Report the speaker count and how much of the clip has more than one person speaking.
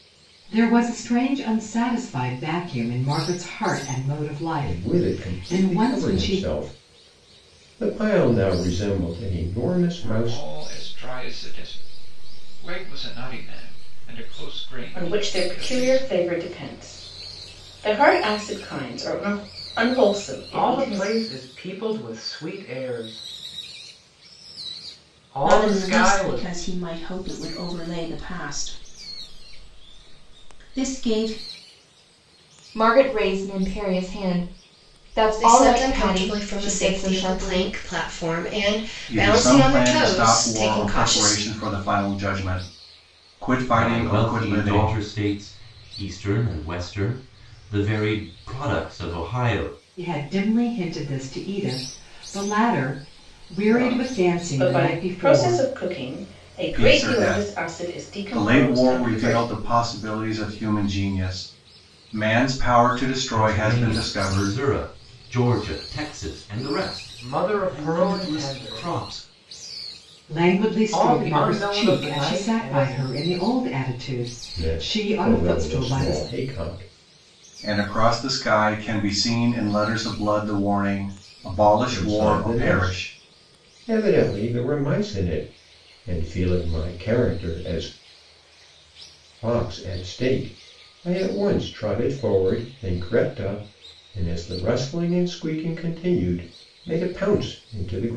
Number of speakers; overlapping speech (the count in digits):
10, about 25%